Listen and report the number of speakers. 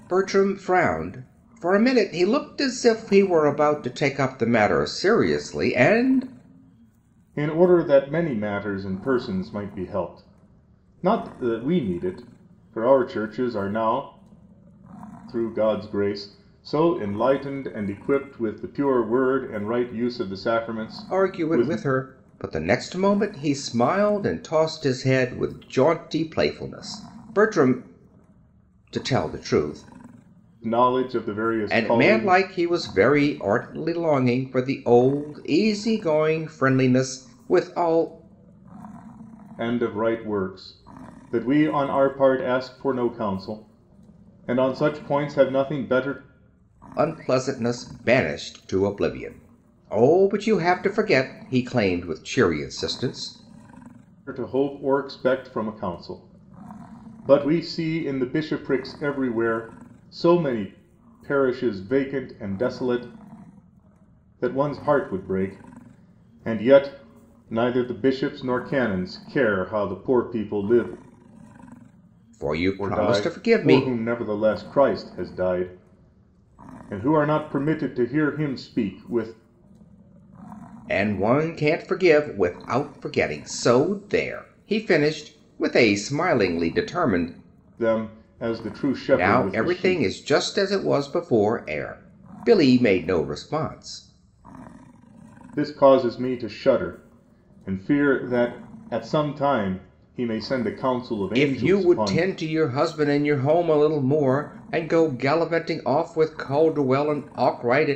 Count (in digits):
2